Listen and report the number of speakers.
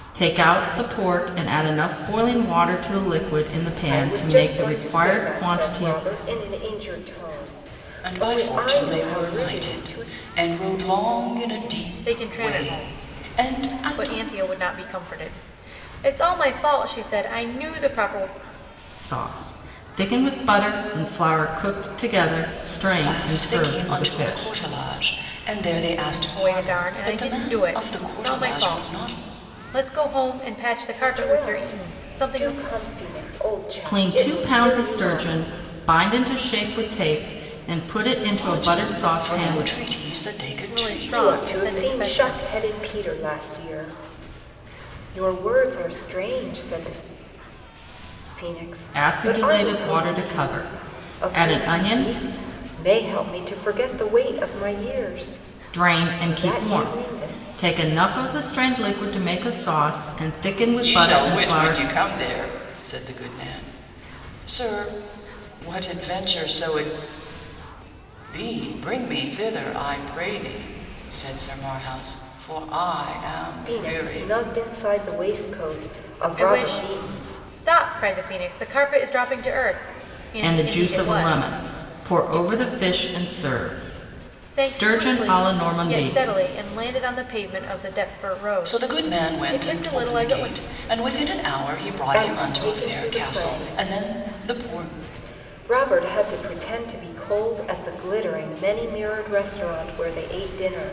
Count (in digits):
4